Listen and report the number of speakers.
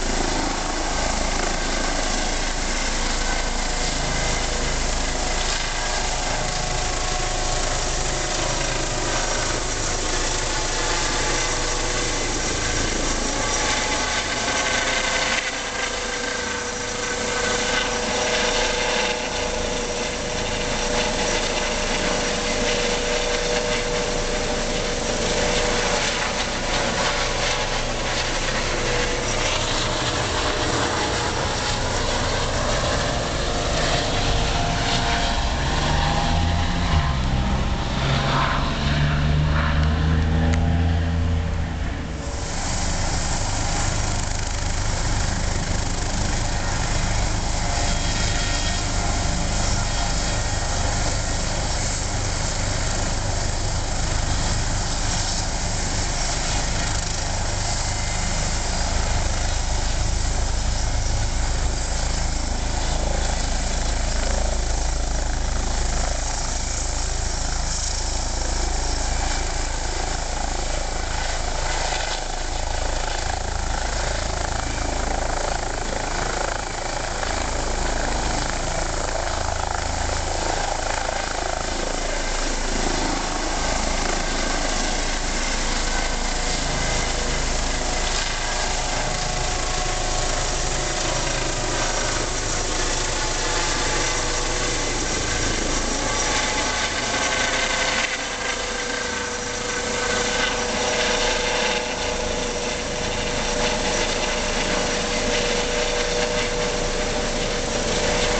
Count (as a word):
zero